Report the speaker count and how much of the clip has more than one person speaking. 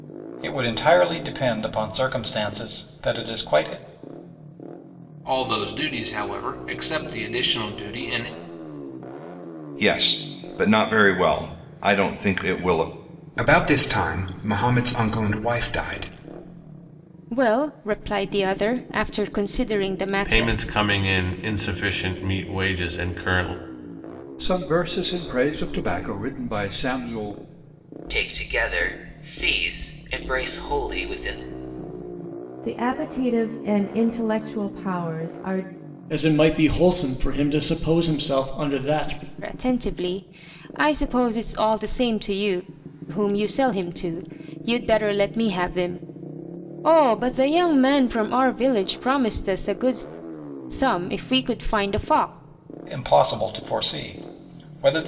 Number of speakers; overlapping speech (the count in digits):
10, about 1%